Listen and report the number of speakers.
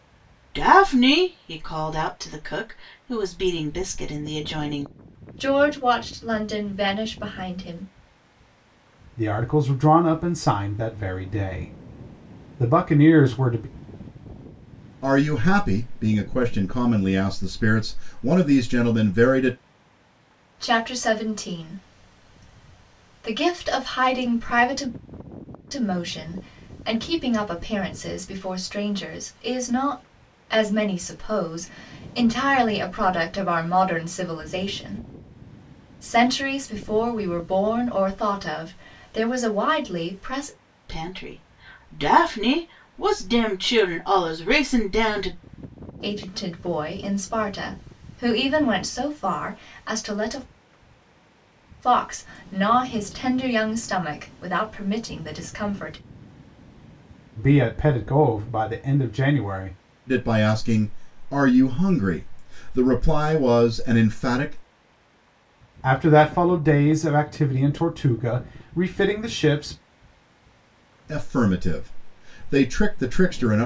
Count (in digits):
4